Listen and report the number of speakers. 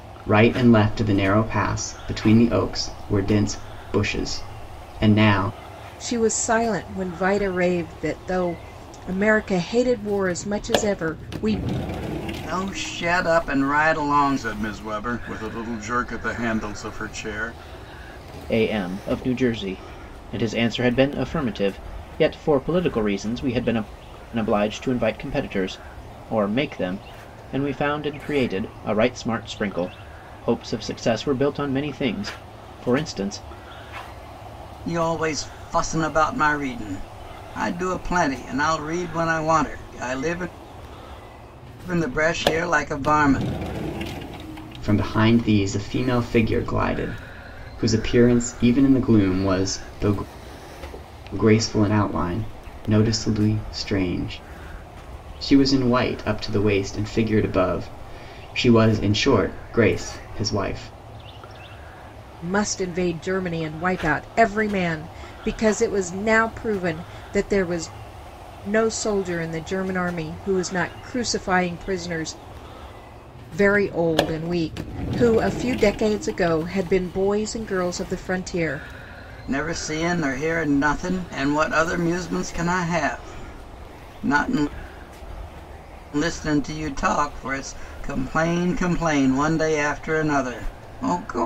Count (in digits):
4